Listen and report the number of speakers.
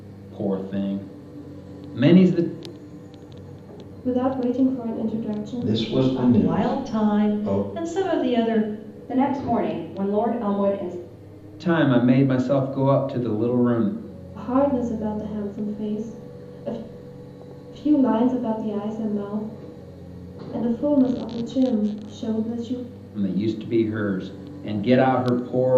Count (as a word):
five